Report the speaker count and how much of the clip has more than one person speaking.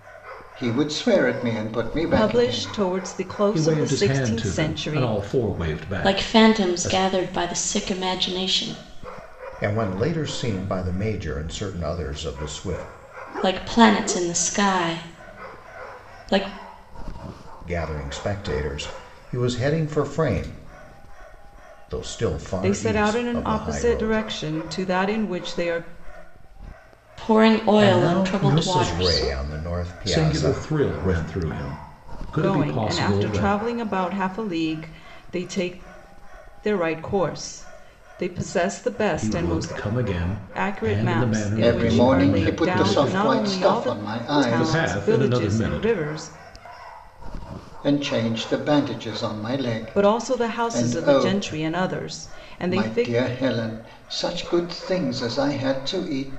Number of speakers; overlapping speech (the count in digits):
5, about 30%